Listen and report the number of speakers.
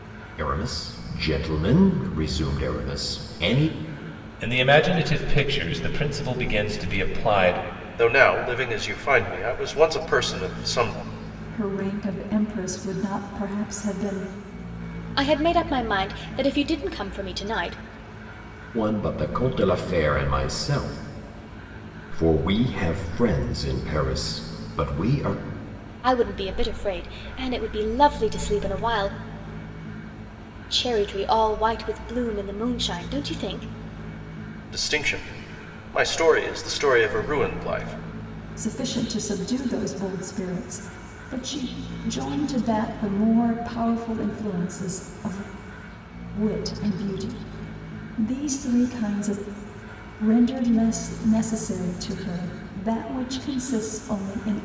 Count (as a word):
five